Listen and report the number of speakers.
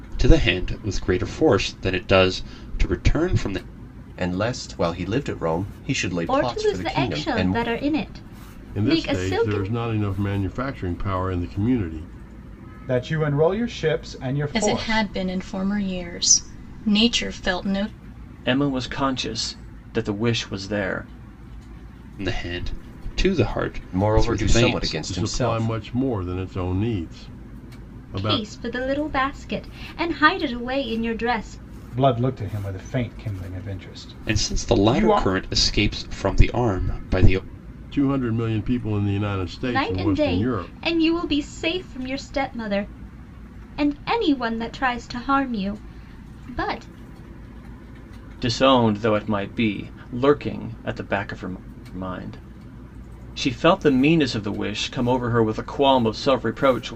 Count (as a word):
seven